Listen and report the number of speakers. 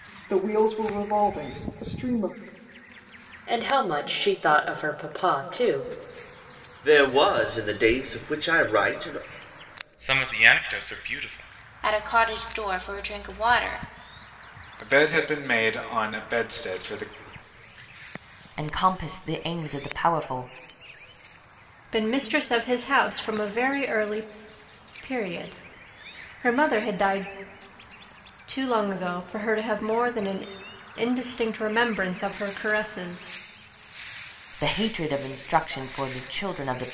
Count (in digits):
8